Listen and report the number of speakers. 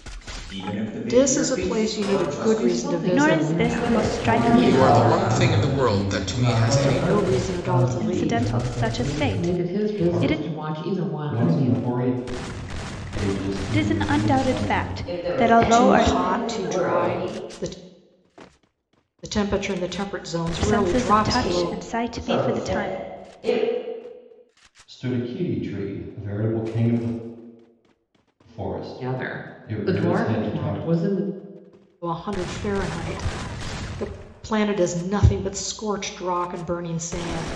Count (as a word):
eight